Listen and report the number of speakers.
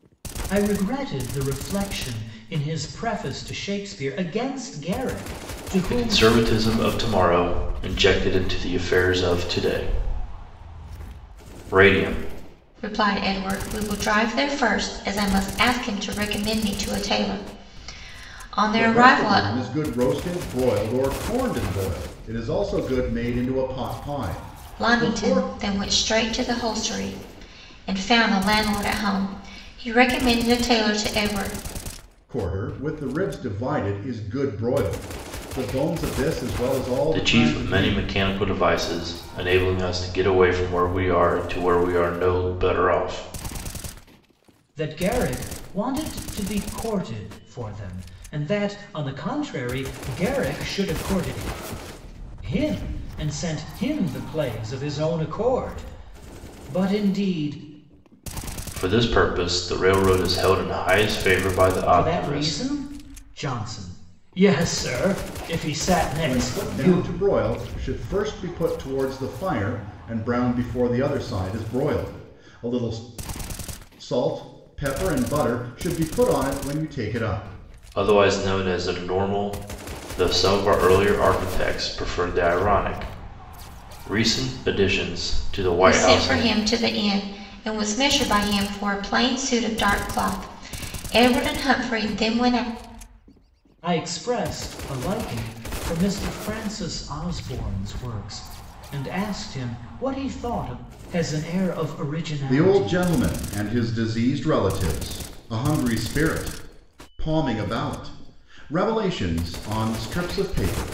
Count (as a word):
four